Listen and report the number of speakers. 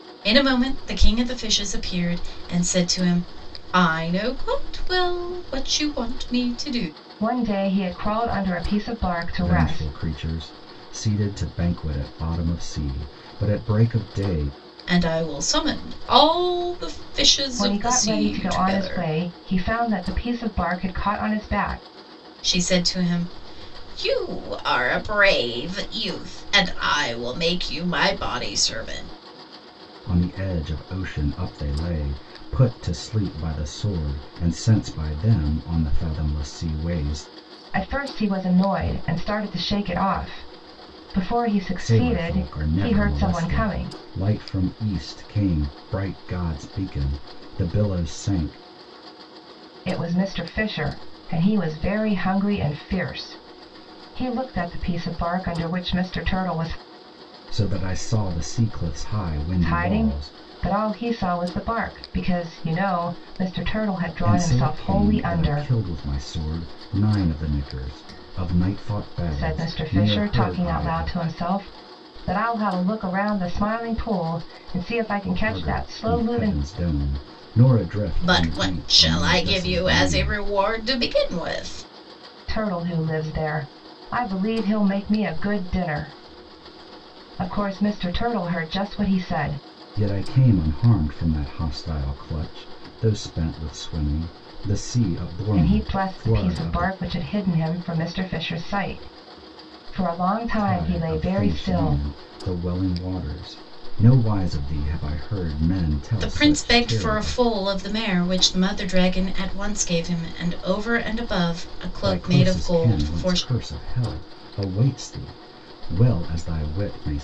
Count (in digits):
3